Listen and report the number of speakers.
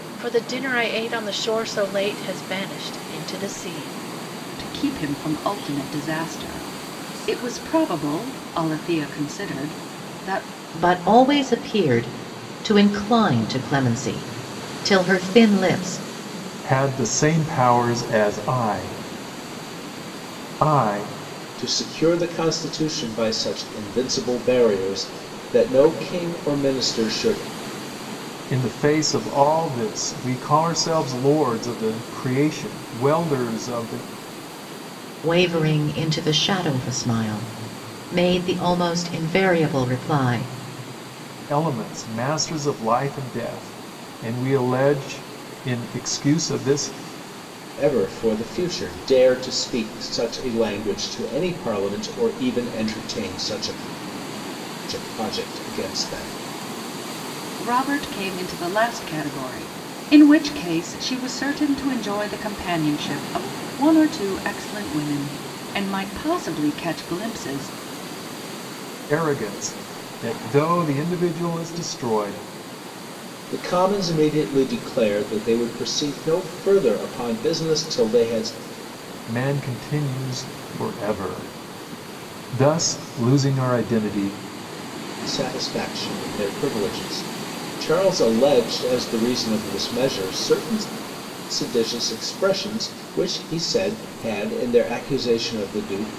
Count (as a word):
five